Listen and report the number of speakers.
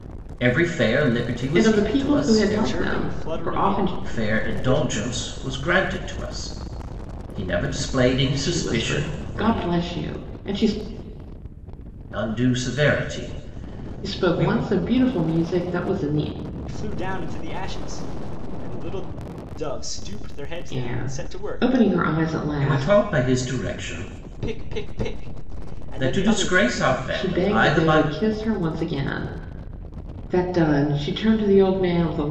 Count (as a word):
three